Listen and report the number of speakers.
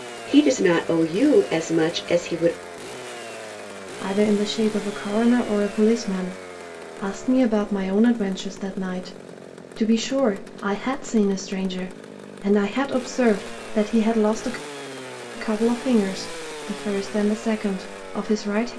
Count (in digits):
2